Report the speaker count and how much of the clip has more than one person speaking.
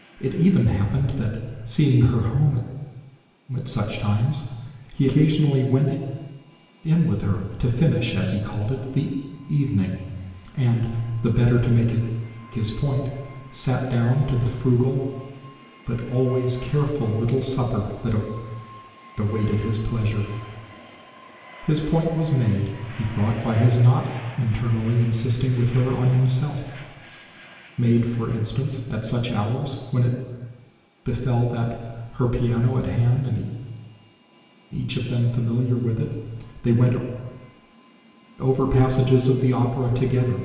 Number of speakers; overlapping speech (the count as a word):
one, no overlap